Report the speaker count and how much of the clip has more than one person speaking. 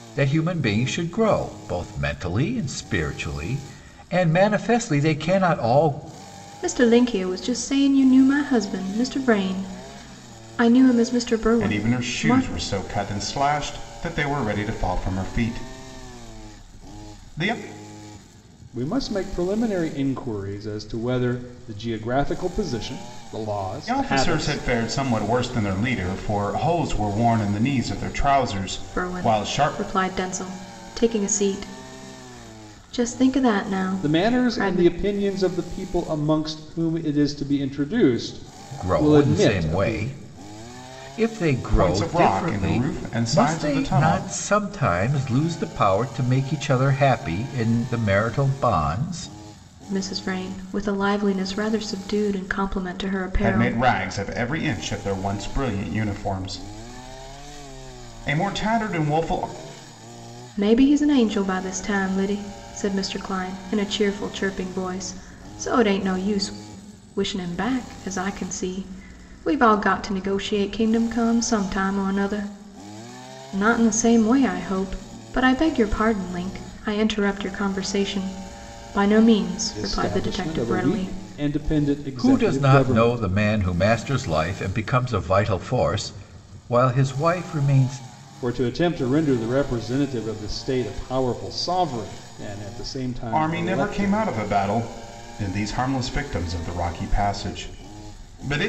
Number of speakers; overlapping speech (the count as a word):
four, about 11%